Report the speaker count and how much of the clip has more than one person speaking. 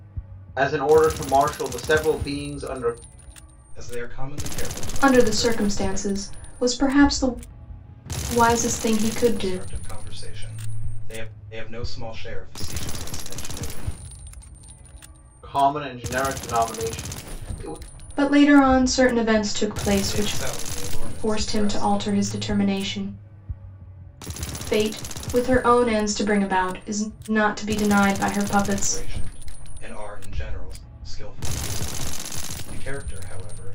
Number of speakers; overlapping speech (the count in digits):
3, about 11%